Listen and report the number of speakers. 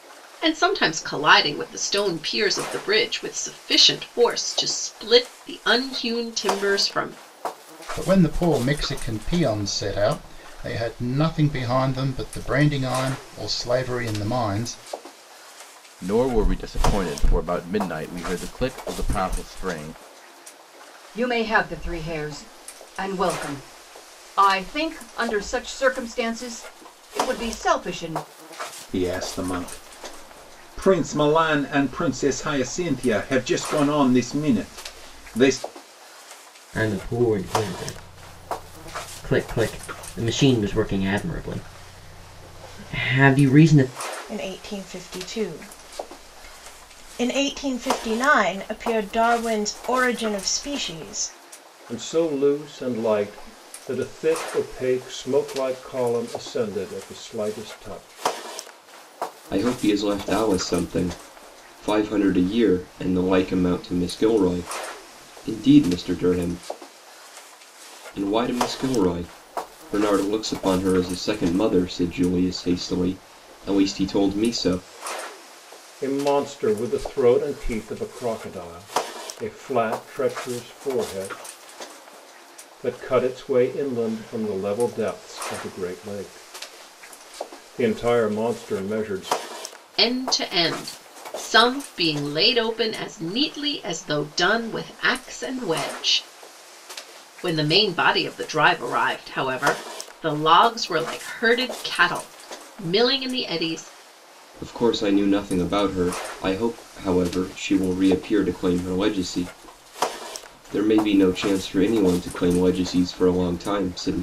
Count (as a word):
nine